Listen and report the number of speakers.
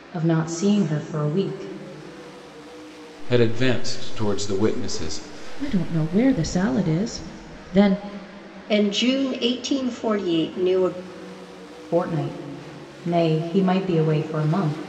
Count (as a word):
four